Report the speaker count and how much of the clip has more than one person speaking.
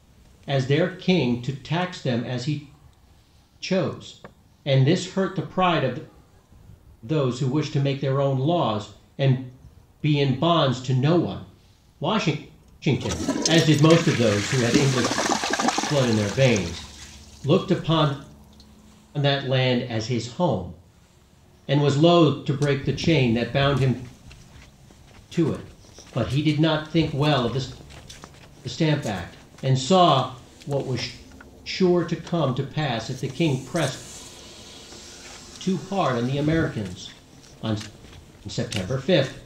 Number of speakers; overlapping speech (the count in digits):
1, no overlap